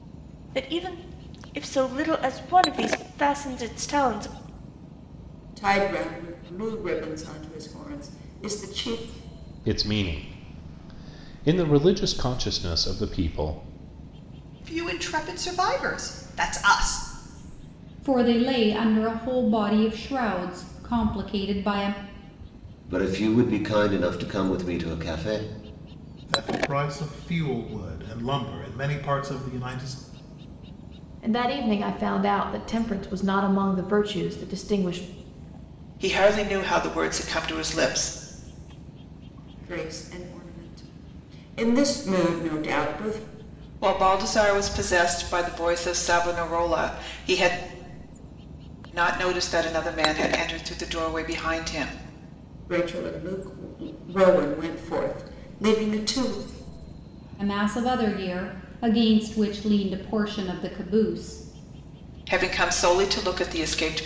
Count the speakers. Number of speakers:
nine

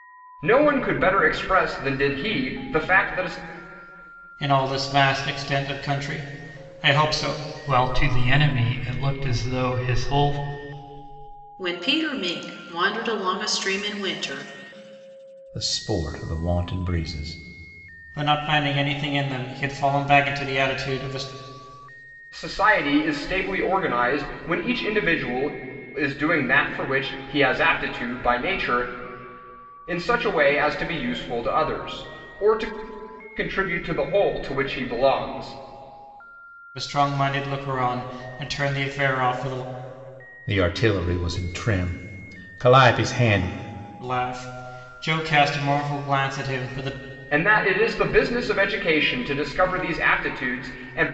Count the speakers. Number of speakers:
five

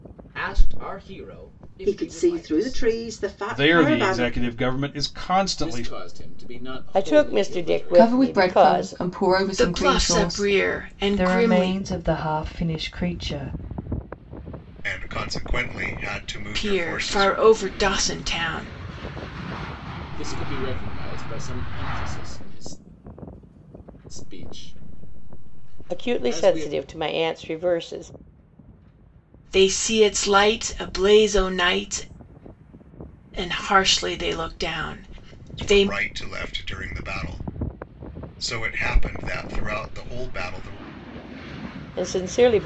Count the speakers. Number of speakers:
nine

